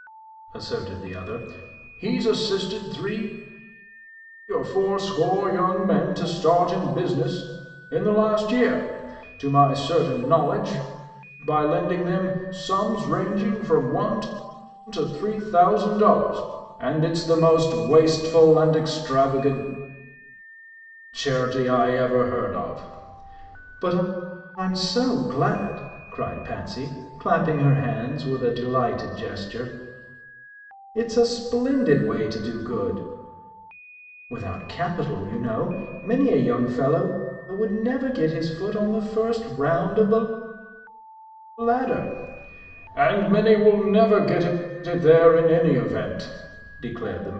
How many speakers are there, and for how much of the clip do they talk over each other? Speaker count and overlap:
1, no overlap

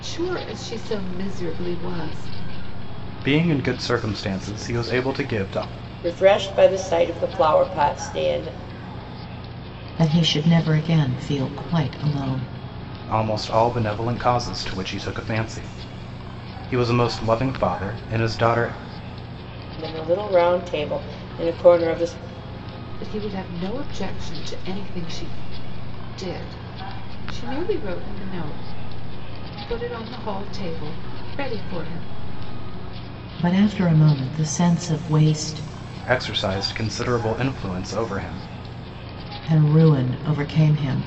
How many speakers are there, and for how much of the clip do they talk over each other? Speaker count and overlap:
4, no overlap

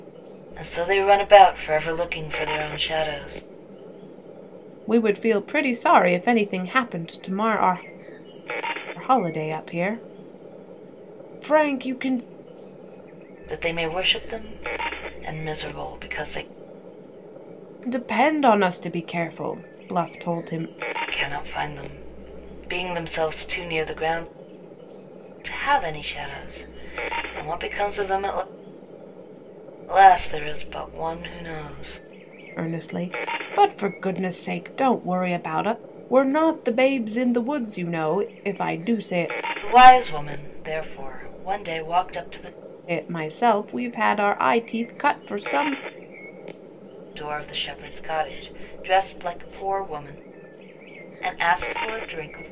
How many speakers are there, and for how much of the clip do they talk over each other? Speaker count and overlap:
2, no overlap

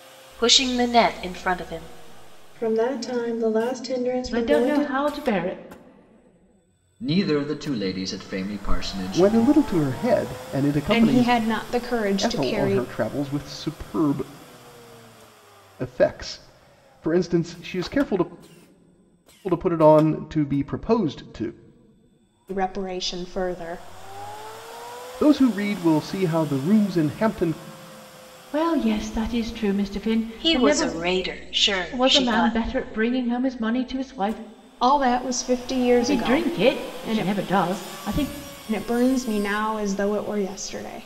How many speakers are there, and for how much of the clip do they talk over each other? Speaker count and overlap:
6, about 12%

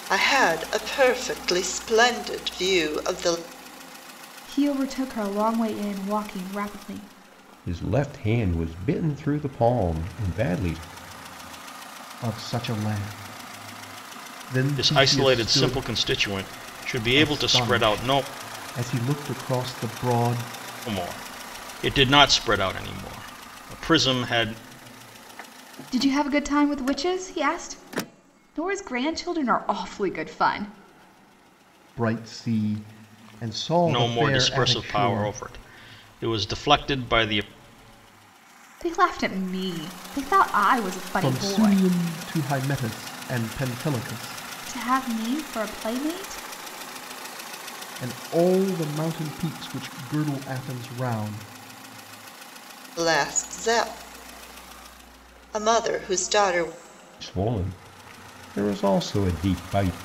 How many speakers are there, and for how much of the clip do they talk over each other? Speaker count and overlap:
5, about 7%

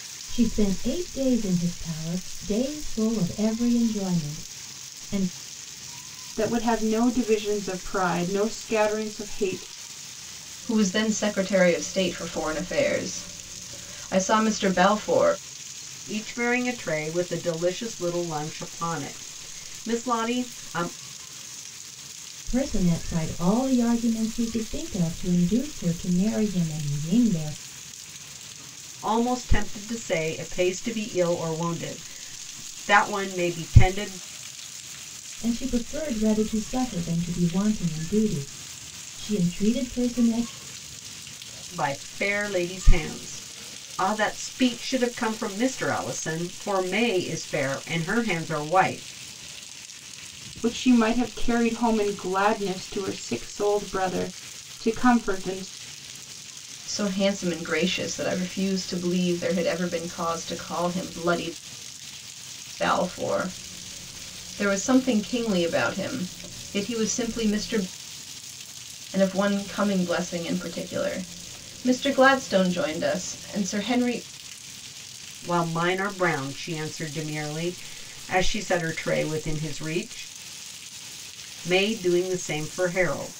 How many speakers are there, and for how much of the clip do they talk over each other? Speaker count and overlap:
4, no overlap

